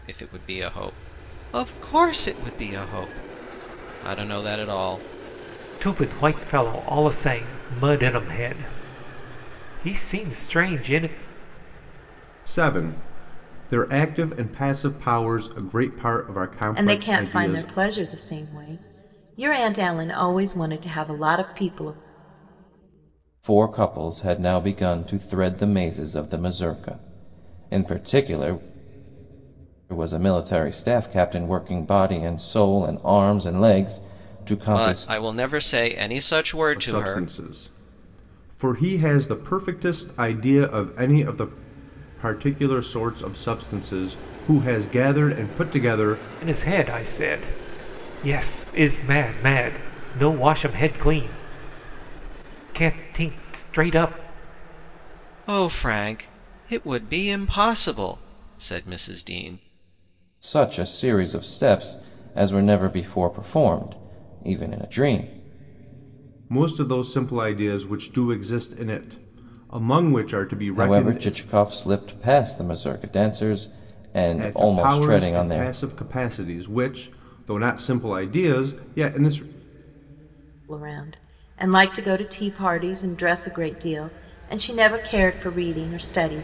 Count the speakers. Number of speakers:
5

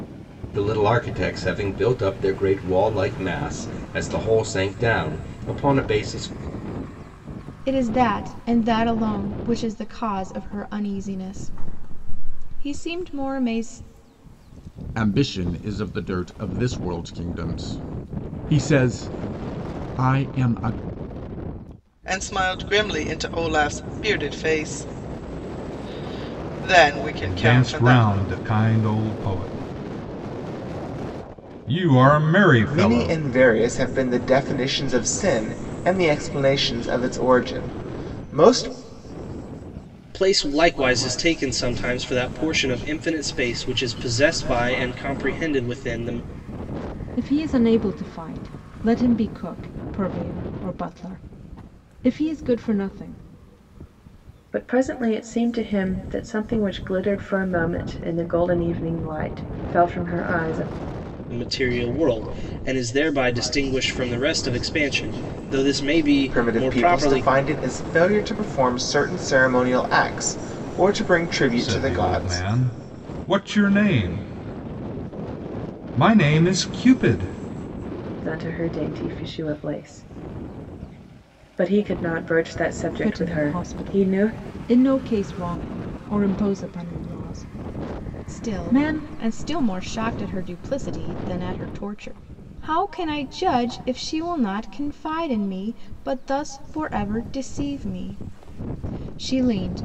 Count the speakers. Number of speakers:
9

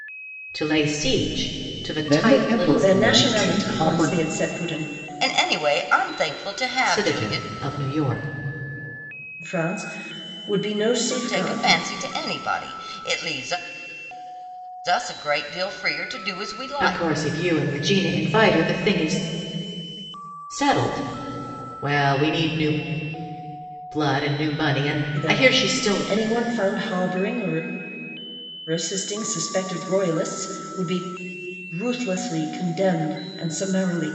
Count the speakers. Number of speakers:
4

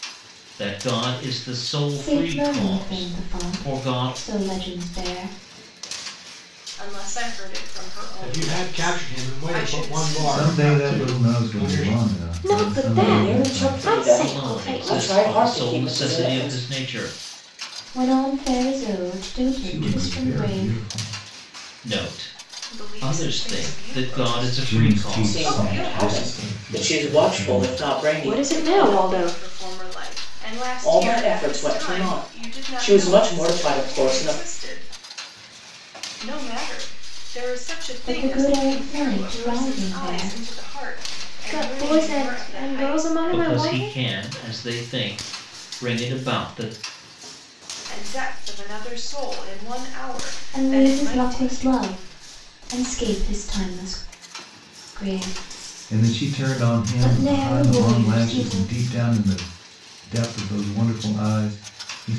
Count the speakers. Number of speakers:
7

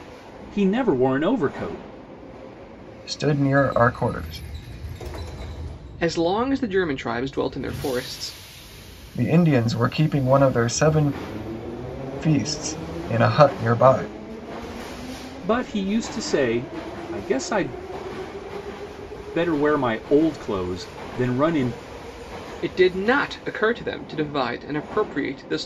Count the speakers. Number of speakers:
3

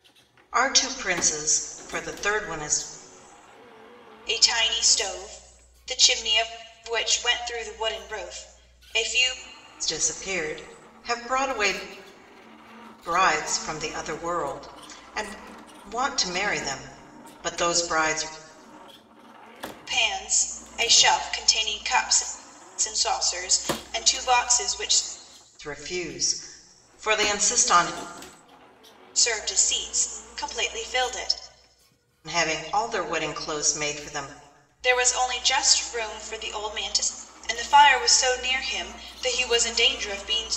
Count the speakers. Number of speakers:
2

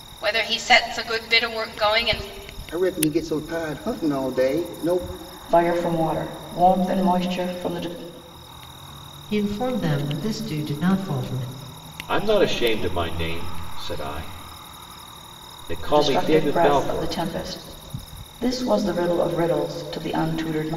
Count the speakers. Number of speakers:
5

